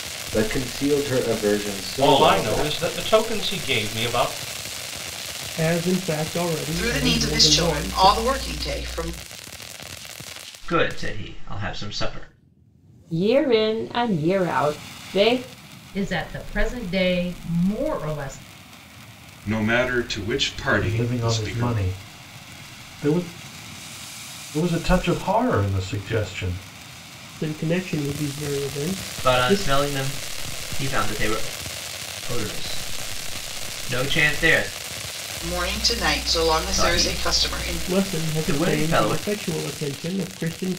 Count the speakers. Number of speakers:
9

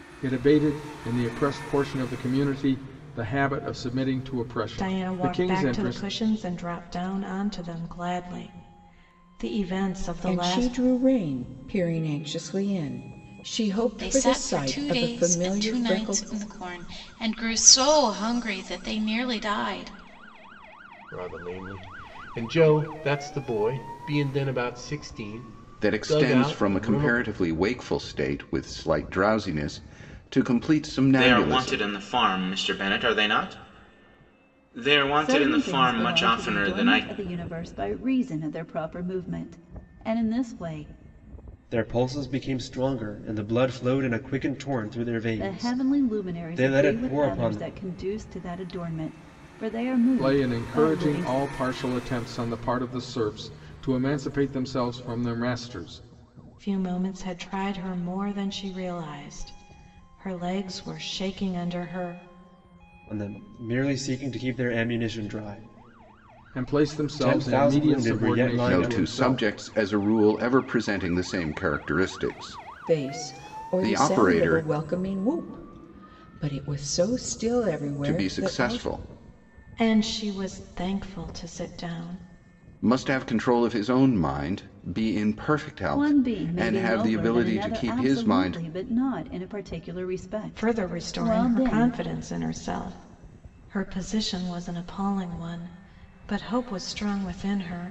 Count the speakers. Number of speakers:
9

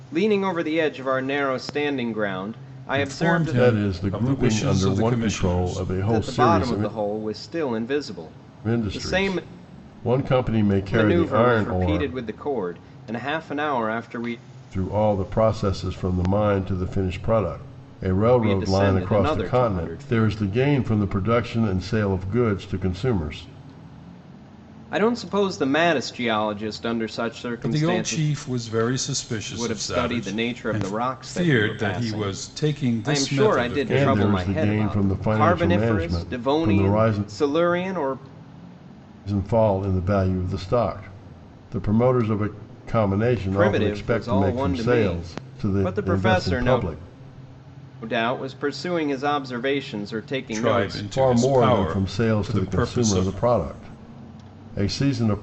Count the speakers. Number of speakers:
3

